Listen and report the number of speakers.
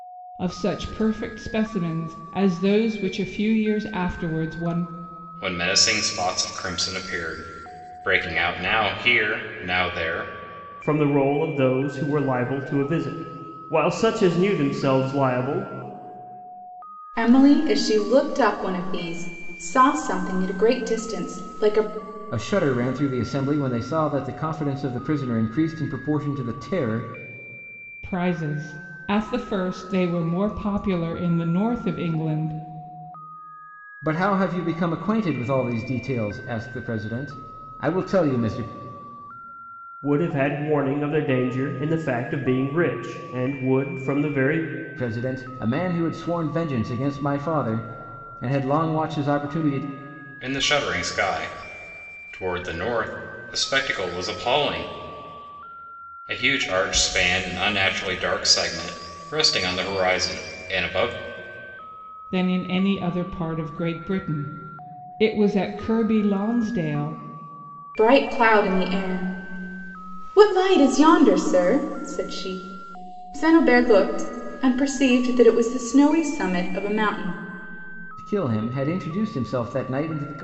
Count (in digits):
5